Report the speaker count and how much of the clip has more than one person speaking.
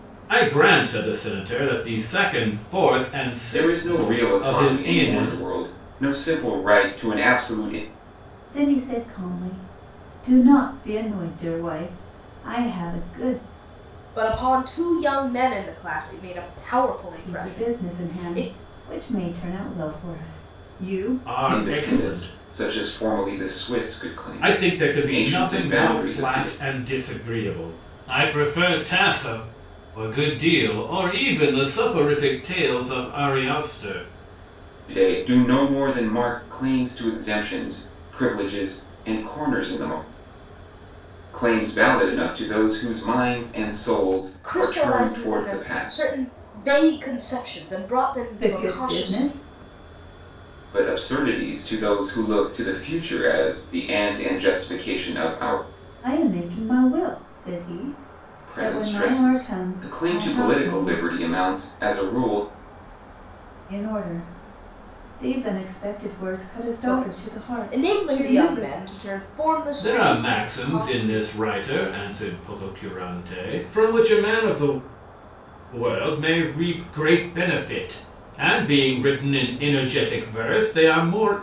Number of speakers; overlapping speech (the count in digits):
4, about 19%